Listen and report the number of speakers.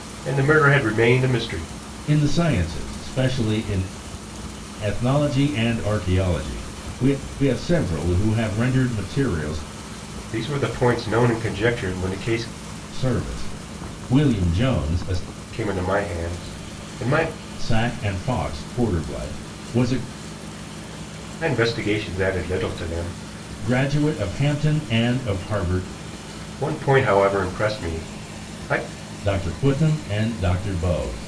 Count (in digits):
2